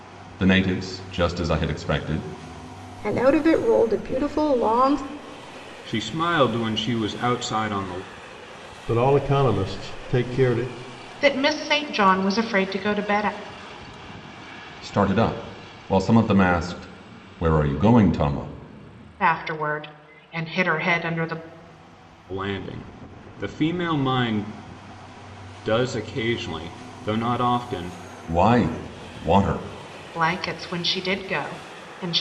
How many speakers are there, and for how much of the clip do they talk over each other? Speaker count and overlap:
five, no overlap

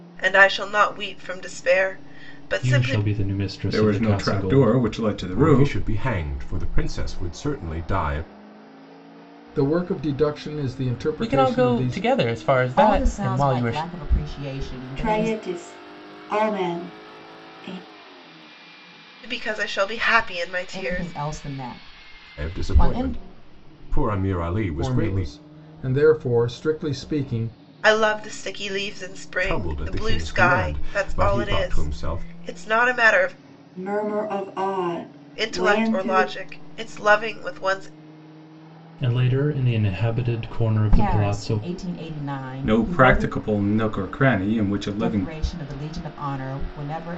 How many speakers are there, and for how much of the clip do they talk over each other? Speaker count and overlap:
eight, about 26%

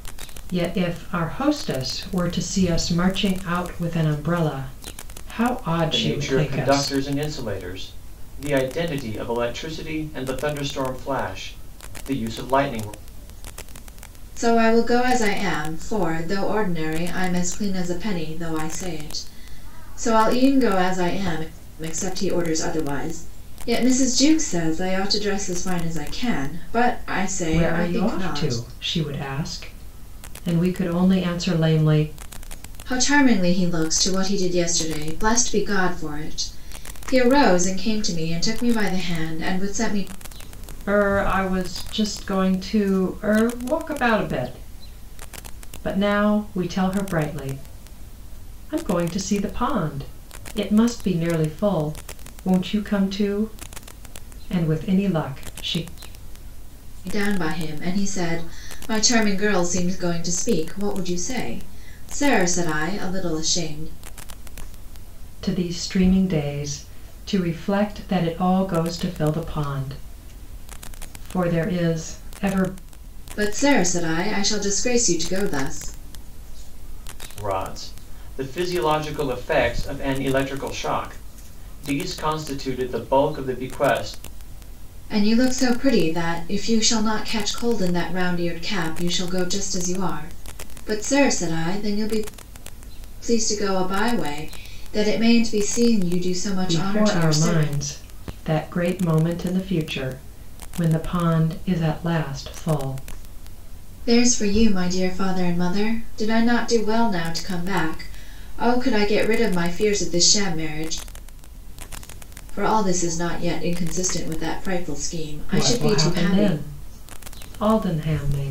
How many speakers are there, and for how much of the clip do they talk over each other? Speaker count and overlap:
three, about 4%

